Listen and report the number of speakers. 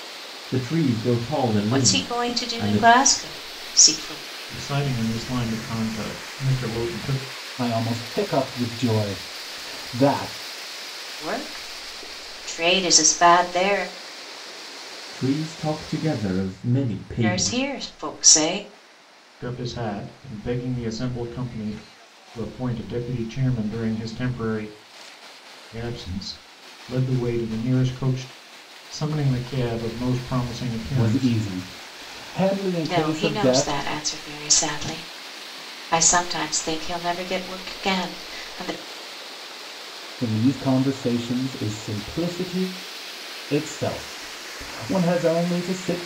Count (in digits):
4